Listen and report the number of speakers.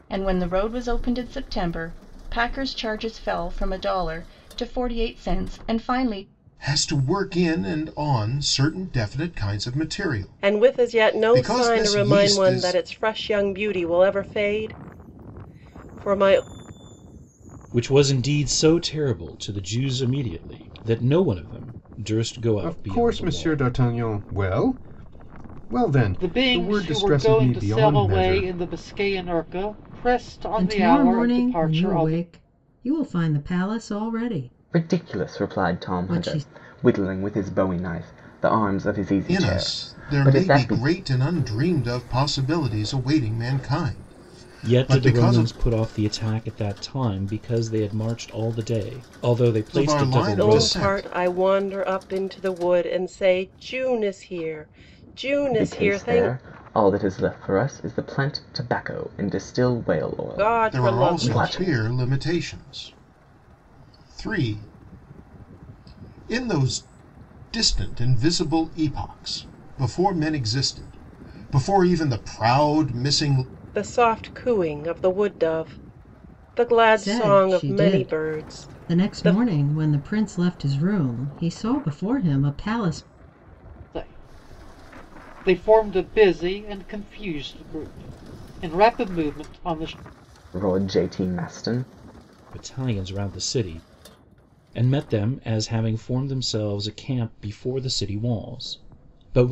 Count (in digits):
8